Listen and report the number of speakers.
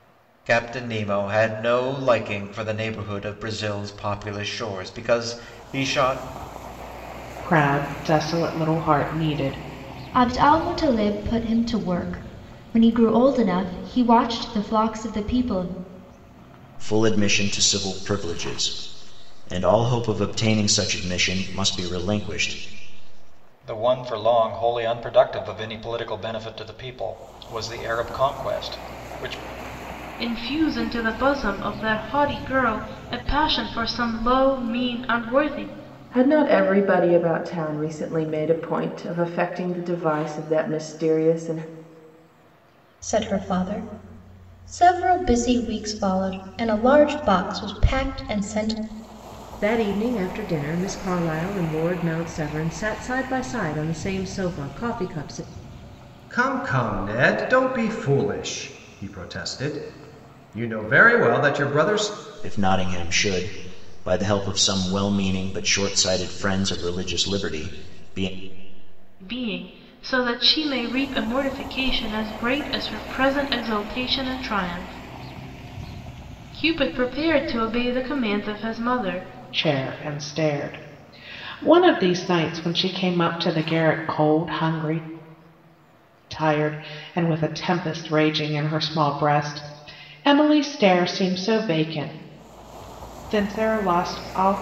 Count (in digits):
10